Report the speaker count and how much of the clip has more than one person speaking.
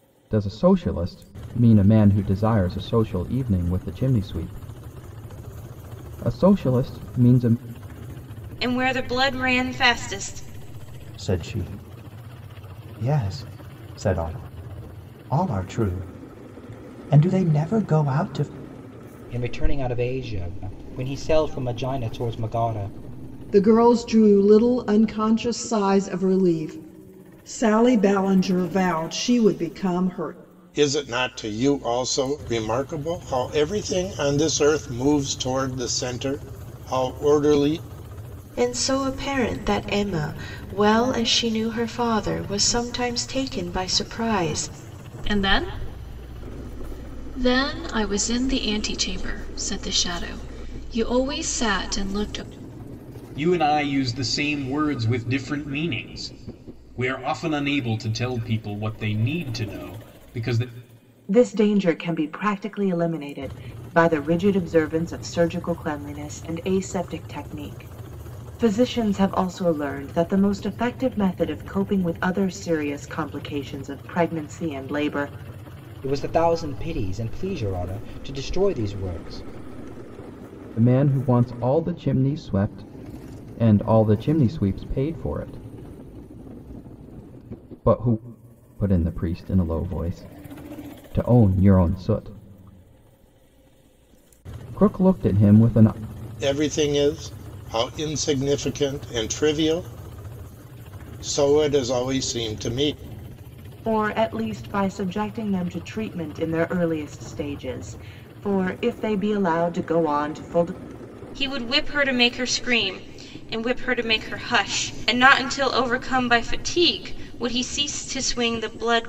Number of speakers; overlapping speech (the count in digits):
10, no overlap